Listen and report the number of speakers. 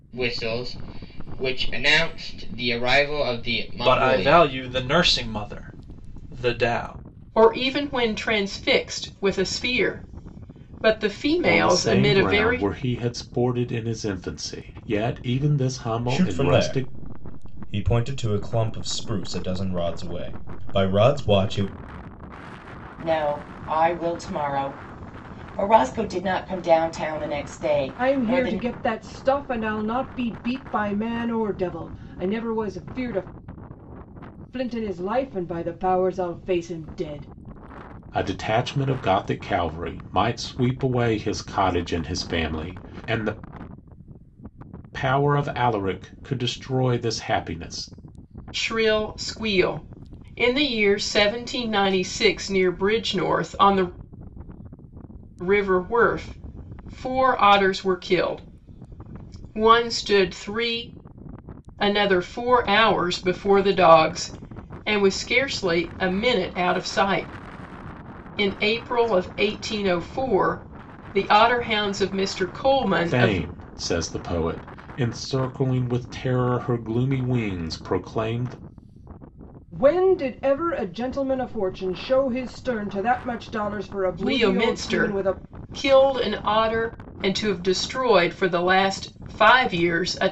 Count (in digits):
7